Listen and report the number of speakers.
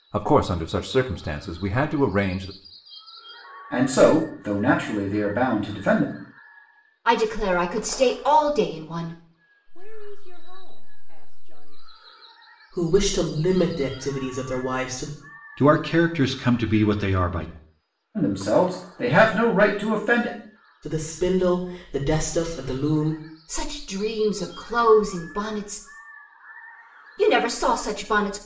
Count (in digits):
6